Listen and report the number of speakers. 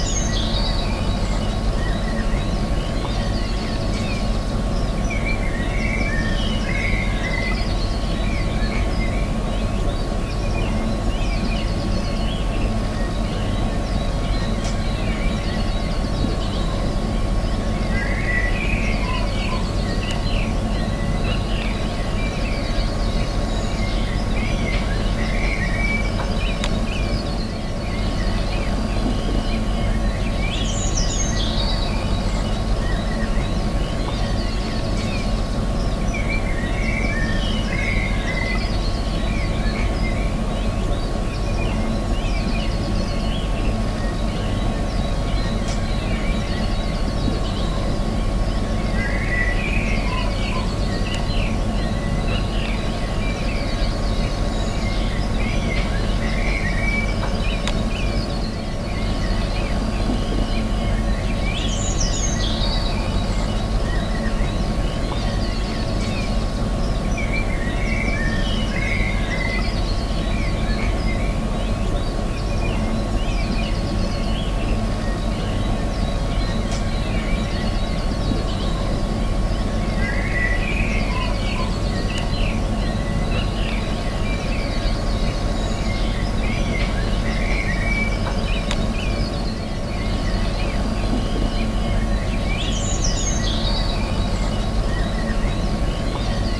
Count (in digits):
0